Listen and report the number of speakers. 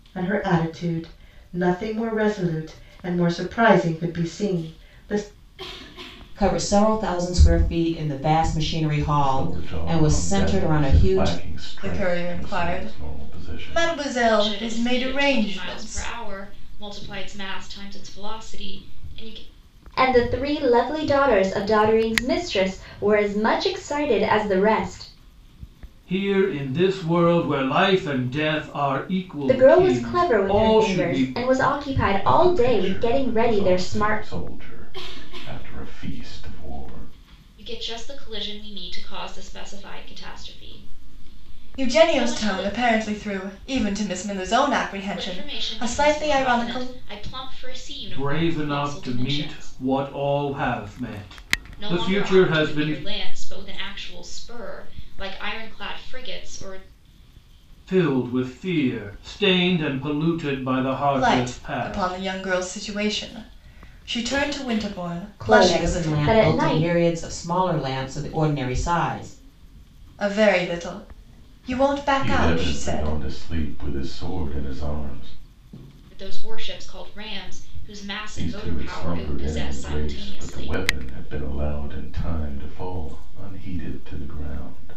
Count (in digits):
7